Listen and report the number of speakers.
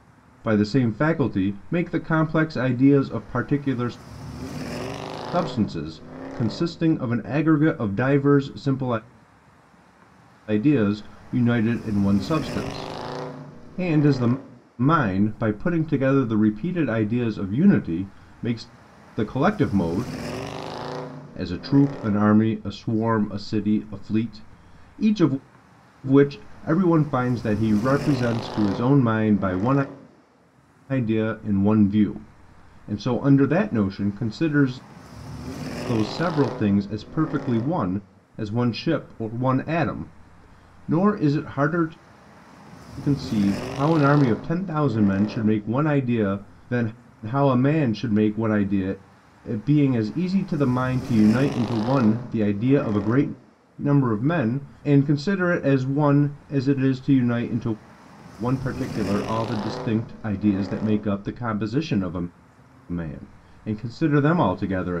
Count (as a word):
one